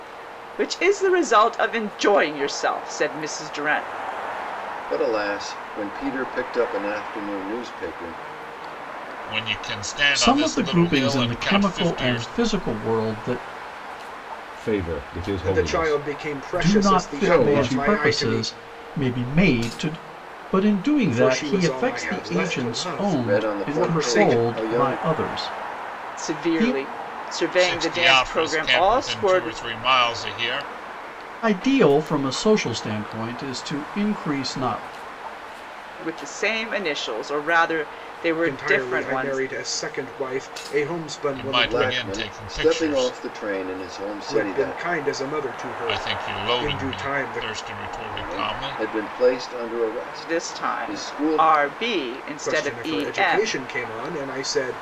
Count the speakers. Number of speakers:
6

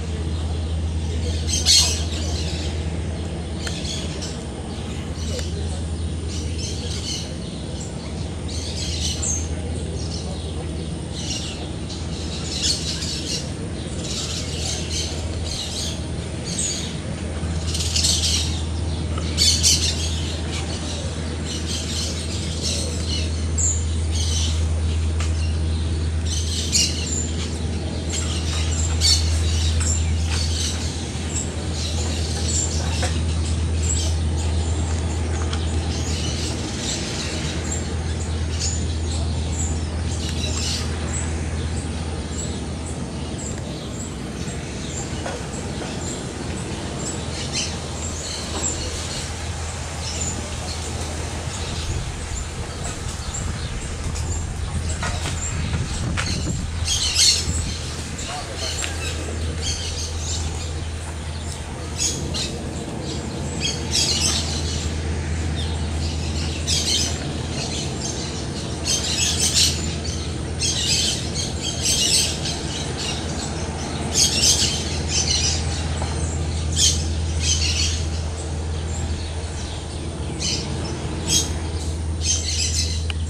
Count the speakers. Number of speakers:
0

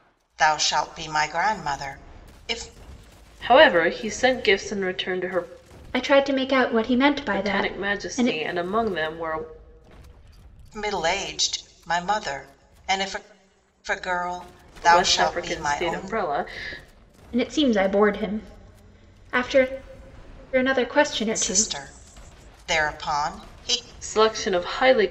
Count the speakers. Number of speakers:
3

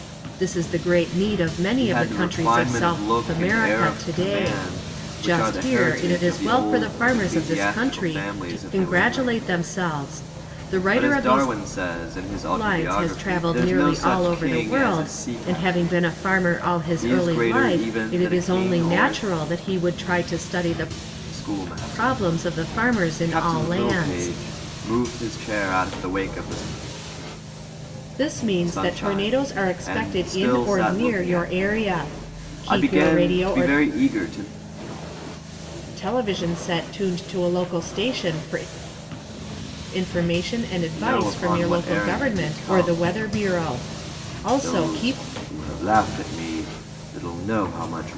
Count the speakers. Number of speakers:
2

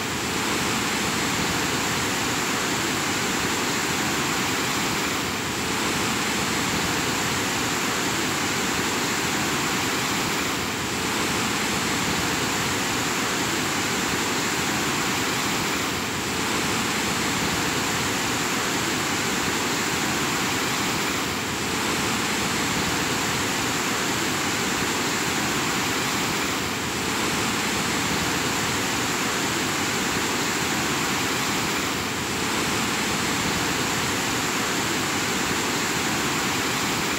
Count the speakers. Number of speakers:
0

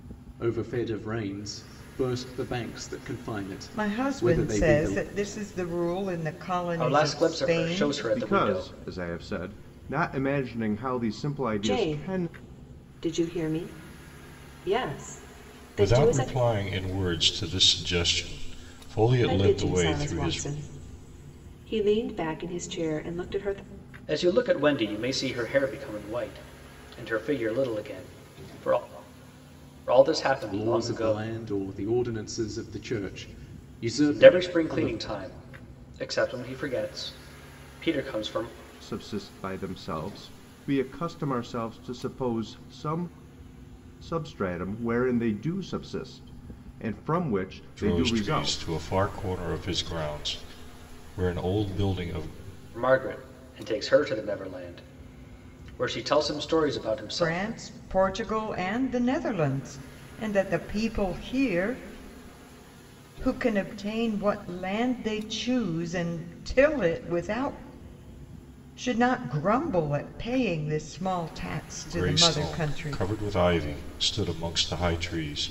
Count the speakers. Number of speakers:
6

